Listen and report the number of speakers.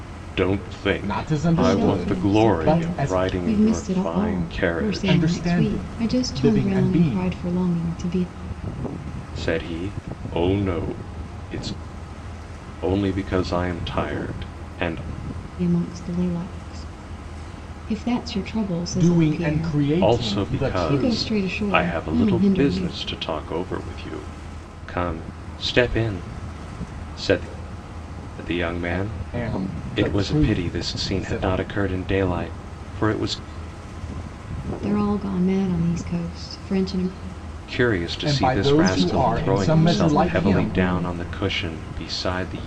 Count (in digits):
3